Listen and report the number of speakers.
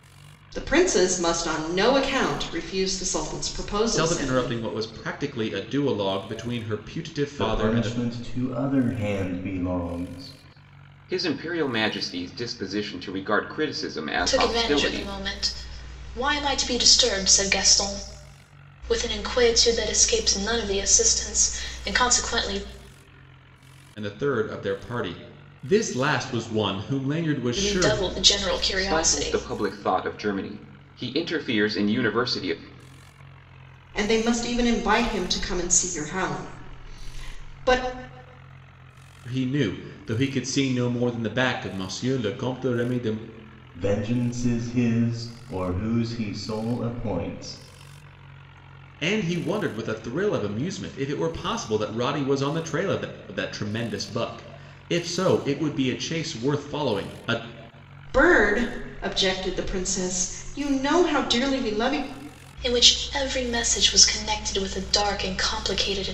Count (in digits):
5